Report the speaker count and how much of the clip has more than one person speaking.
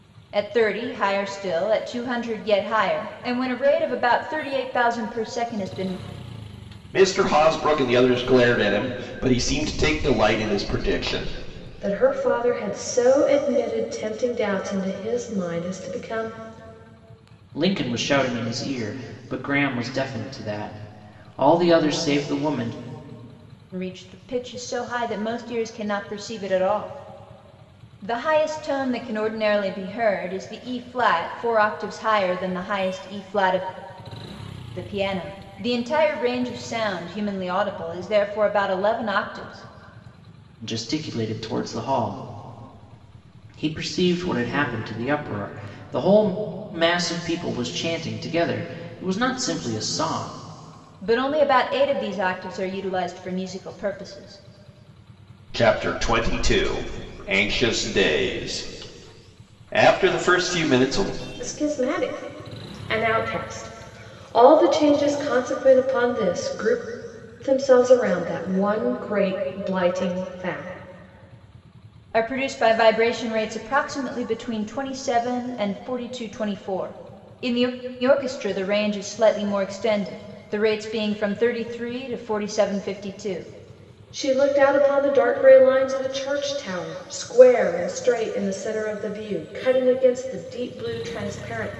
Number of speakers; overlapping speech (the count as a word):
four, no overlap